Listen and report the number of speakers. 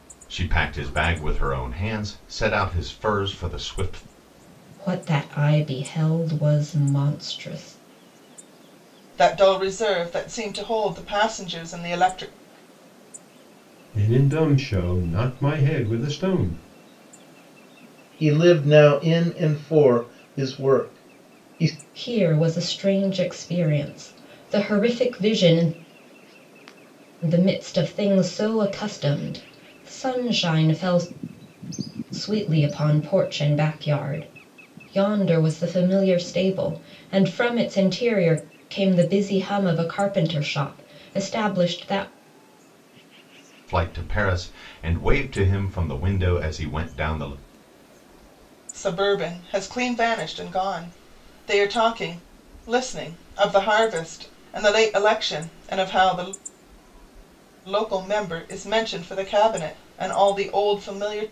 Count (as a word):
five